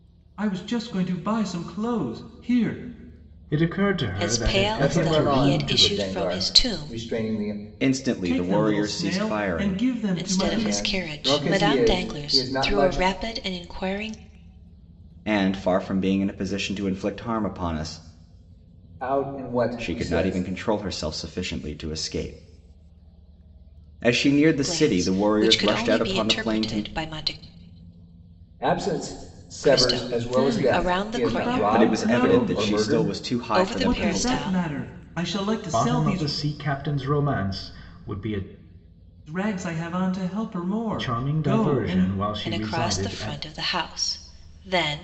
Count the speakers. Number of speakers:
five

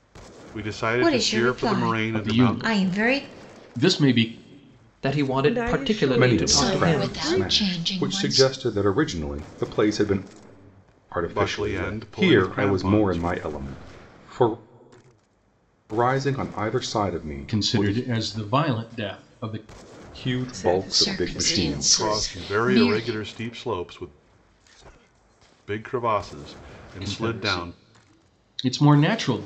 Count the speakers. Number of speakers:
seven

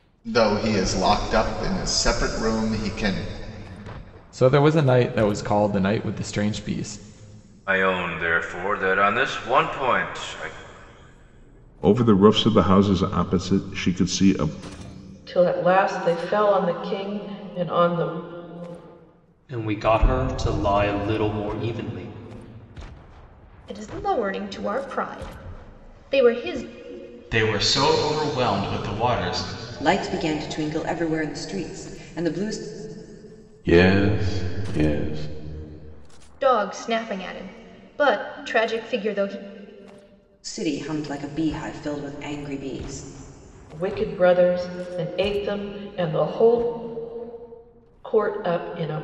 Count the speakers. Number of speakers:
ten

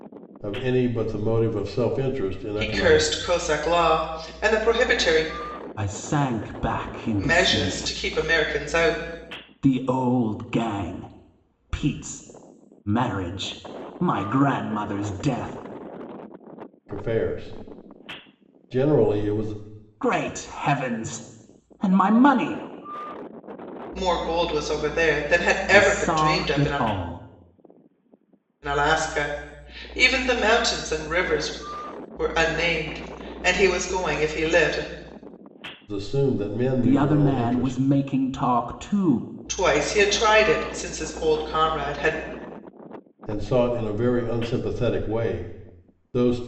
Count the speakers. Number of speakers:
three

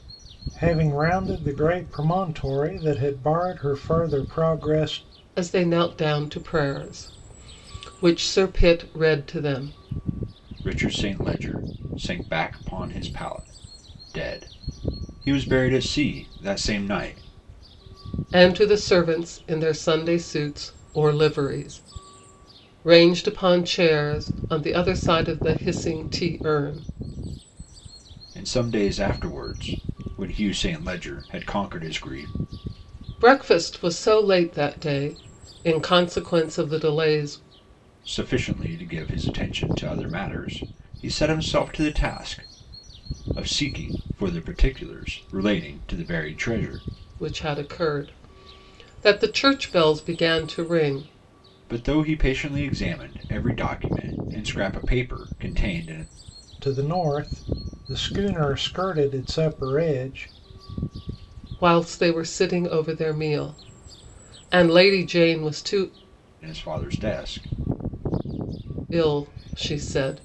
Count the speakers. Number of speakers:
three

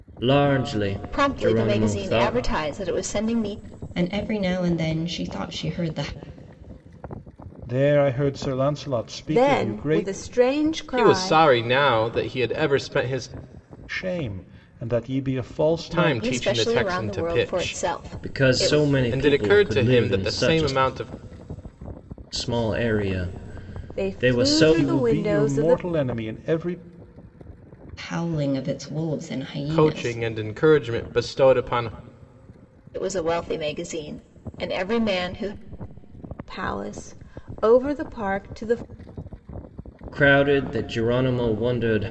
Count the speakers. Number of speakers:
six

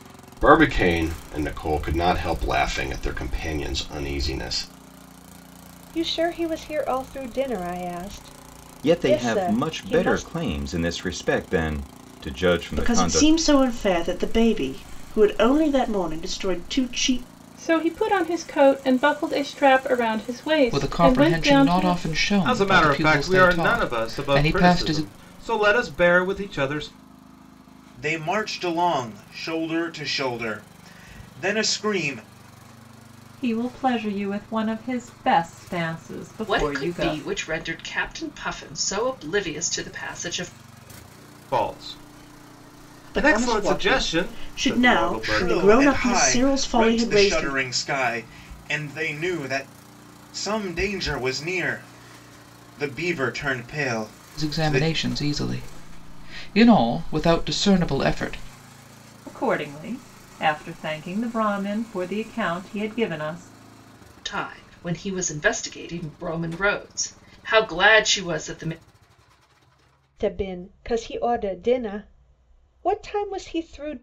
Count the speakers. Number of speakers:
ten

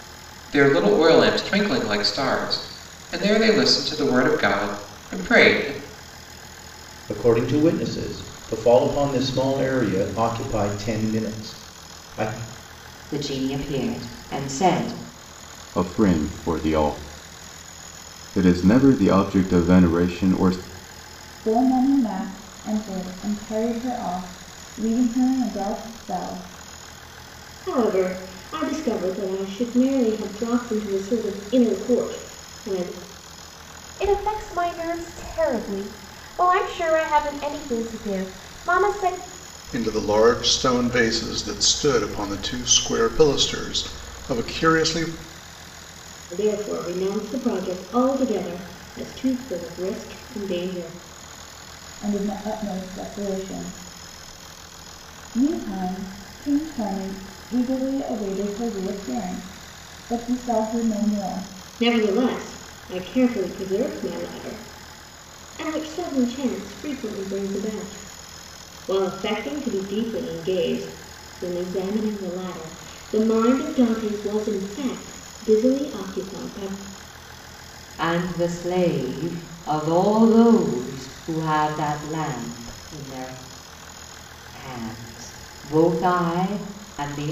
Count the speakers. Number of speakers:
eight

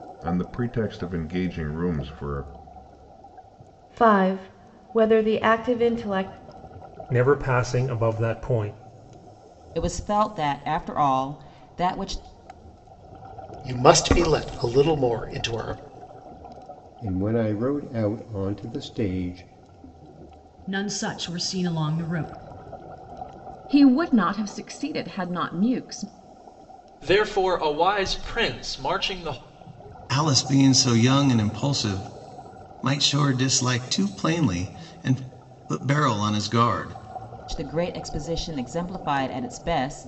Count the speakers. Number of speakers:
ten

